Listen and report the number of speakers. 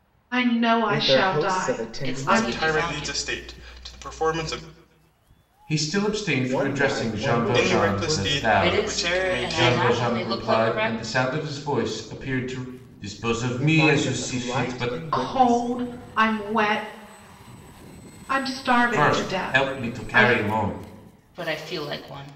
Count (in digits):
5